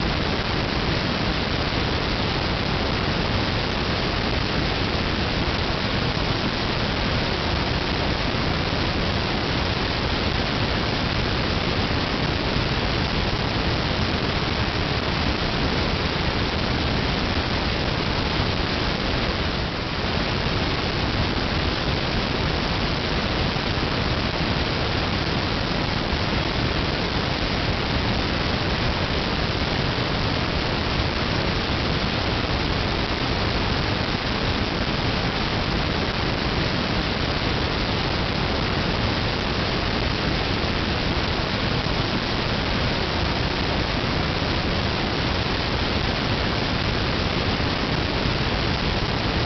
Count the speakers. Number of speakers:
0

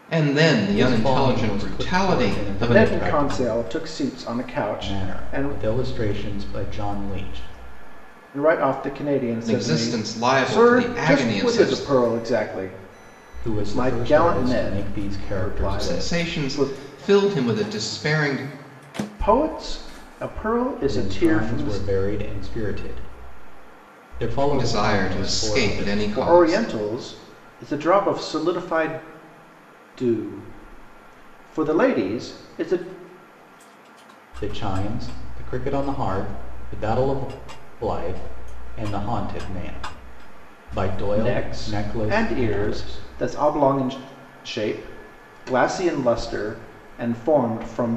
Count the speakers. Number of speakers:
3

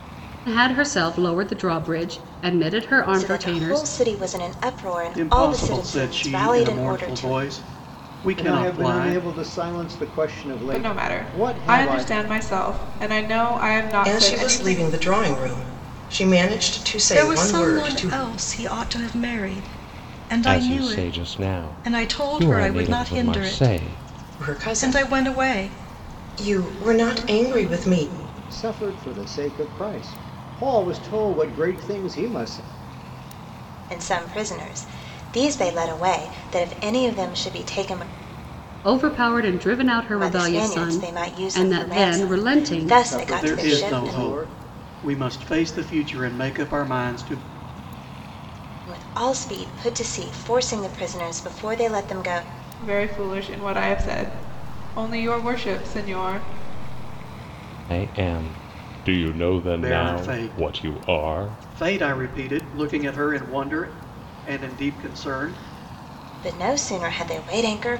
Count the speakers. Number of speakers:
8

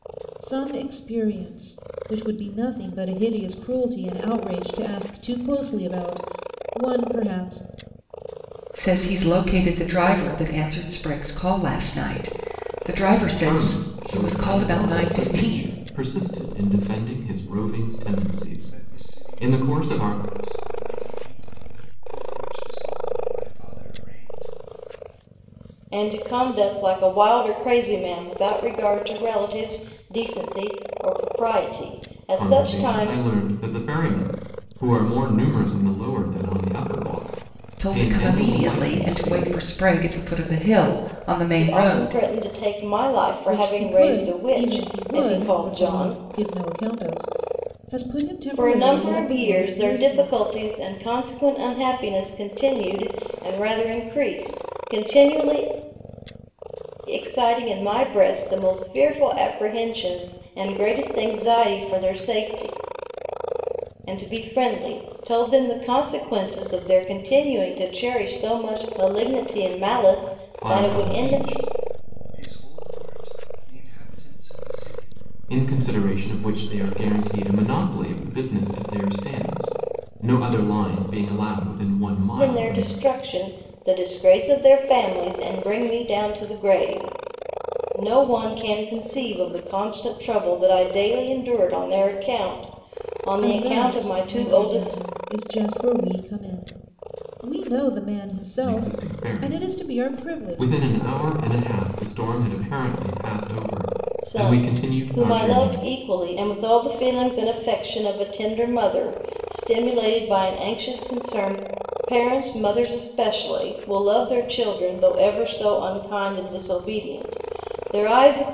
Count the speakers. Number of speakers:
5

